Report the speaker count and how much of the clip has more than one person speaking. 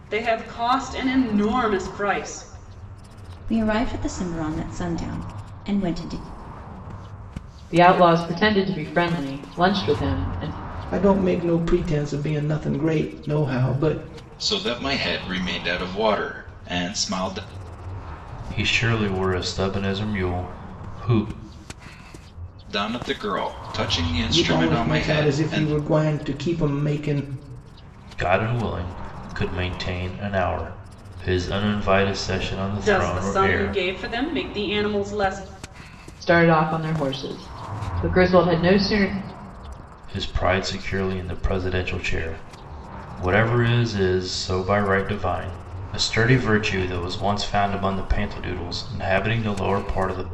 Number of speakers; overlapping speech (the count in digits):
6, about 5%